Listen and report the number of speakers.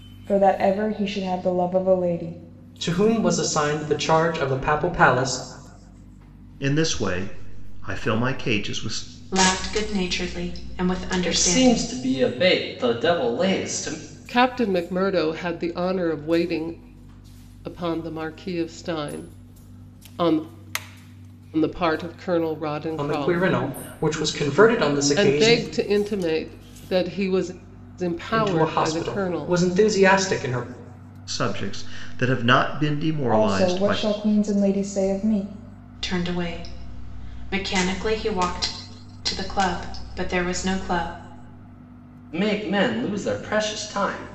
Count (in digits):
6